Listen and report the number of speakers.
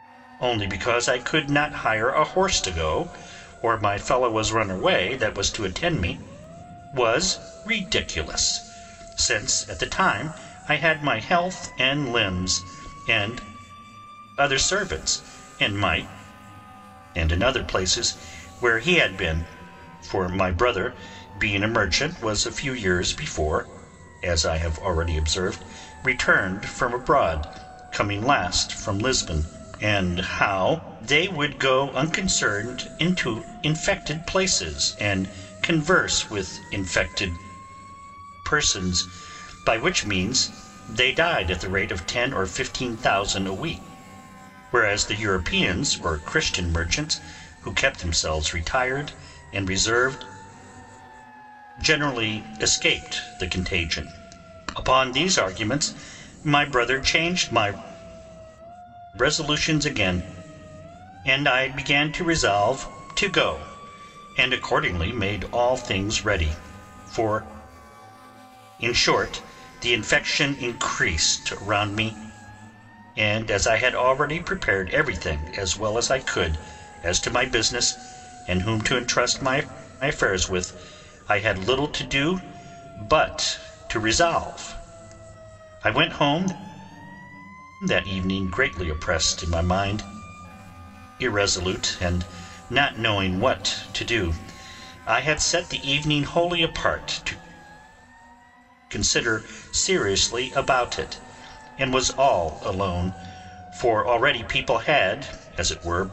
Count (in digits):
1